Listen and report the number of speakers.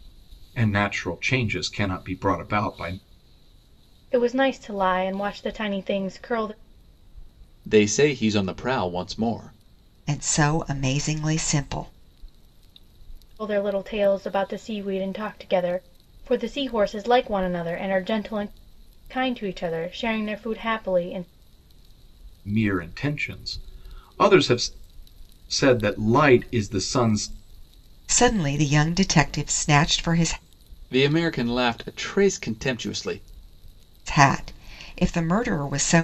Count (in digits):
4